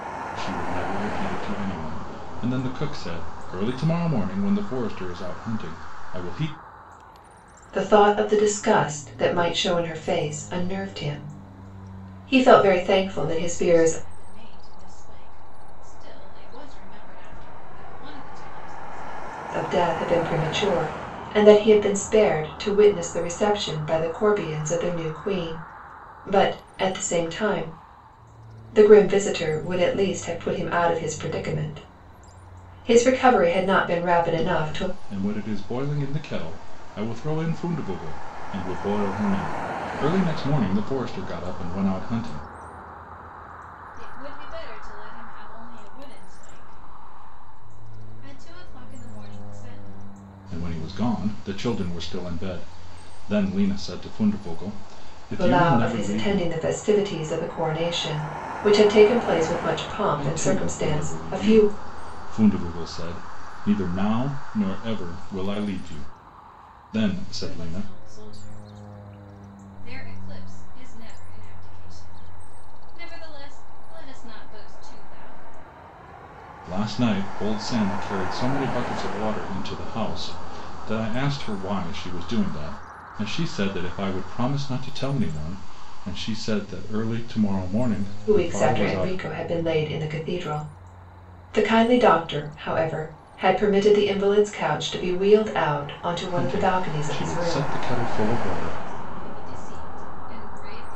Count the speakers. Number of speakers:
3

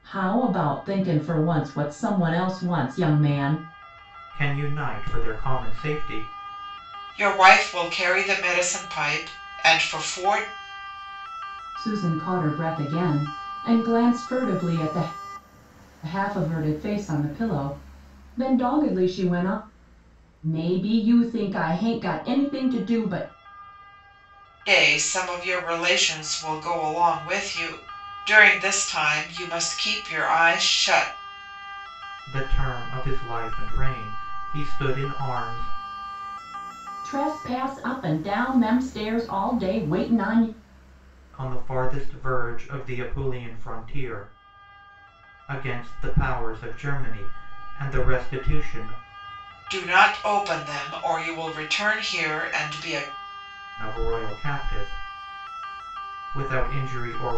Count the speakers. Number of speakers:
3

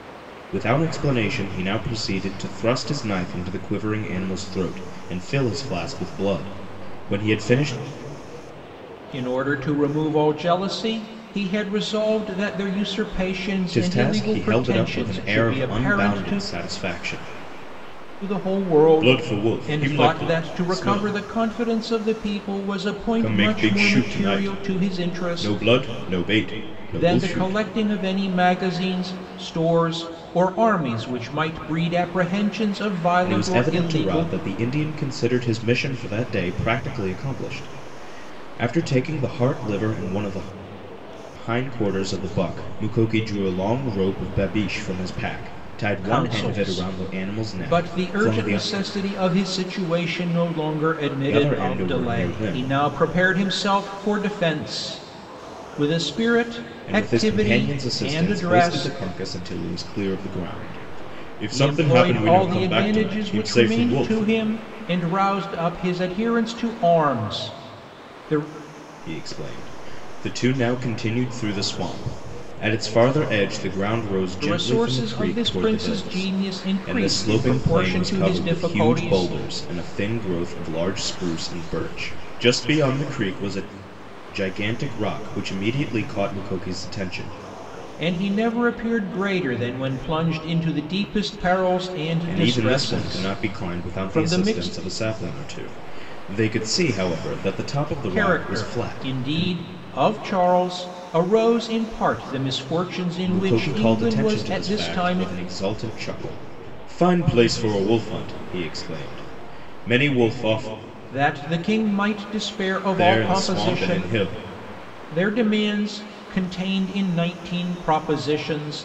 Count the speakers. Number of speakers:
2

